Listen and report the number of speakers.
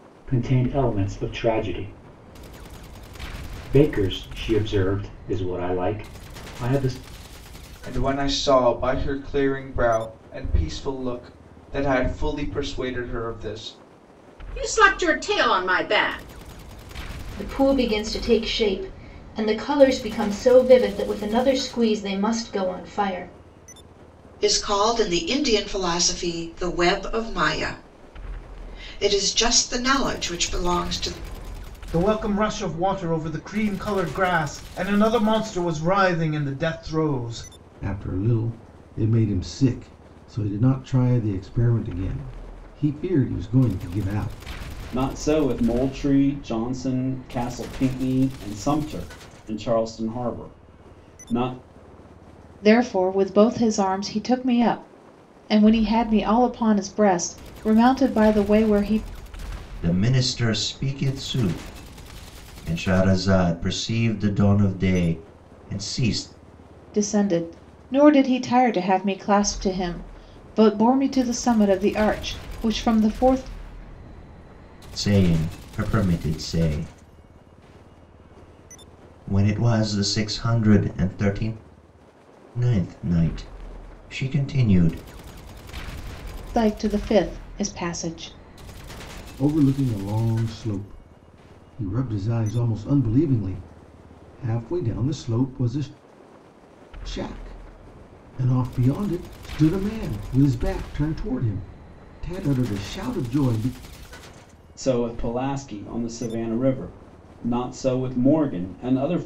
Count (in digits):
10